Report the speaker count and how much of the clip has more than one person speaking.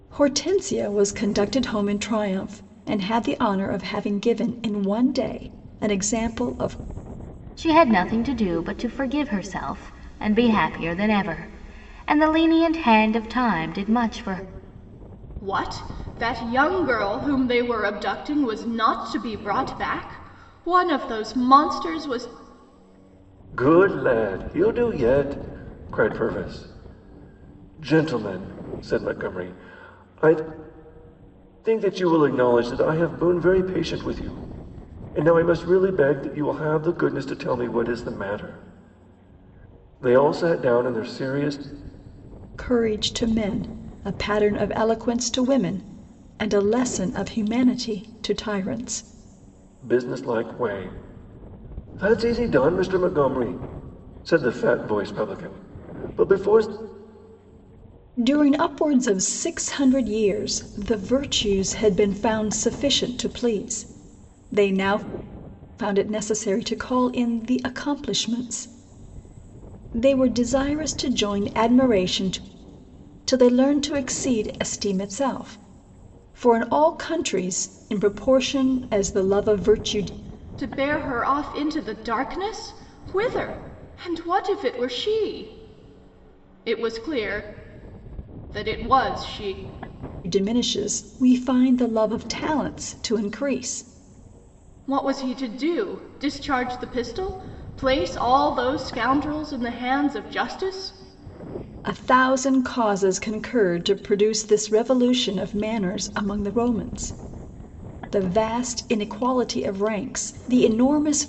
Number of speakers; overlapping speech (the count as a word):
four, no overlap